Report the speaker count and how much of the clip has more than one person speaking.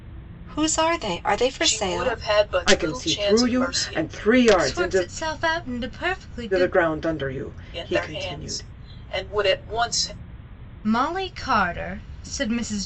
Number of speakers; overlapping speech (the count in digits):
4, about 29%